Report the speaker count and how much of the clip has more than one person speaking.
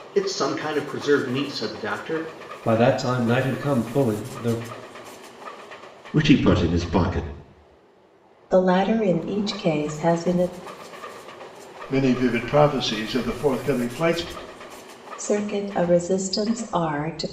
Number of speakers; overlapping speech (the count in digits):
5, no overlap